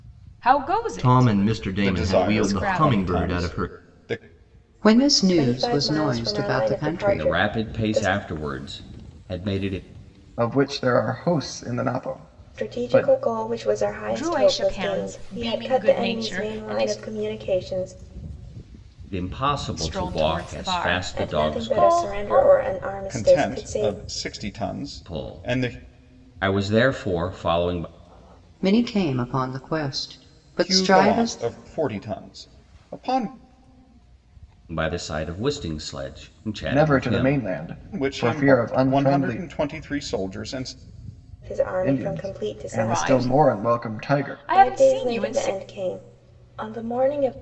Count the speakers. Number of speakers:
7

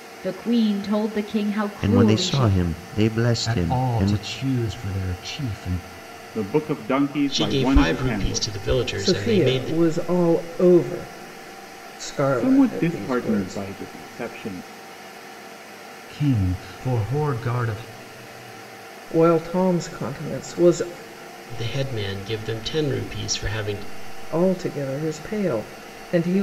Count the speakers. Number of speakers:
6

